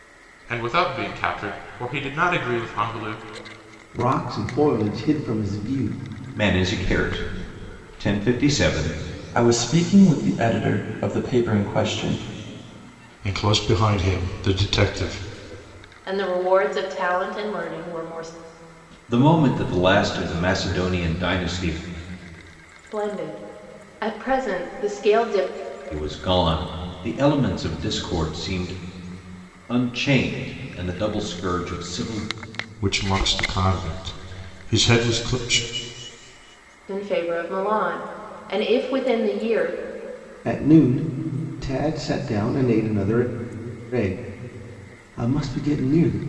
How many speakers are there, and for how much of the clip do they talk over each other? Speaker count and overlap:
six, no overlap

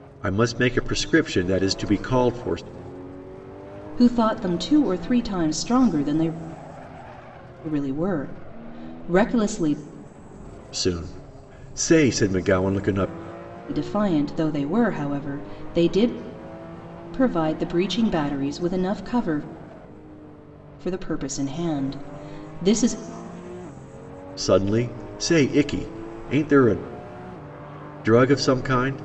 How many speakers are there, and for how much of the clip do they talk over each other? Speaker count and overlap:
two, no overlap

